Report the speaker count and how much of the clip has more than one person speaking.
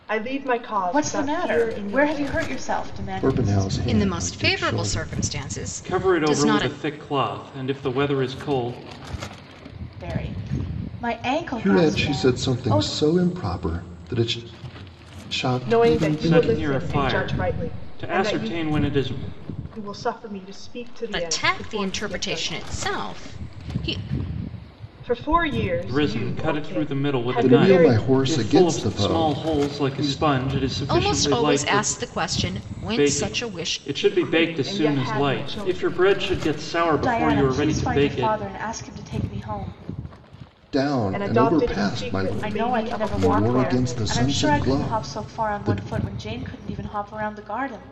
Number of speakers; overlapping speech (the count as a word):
five, about 53%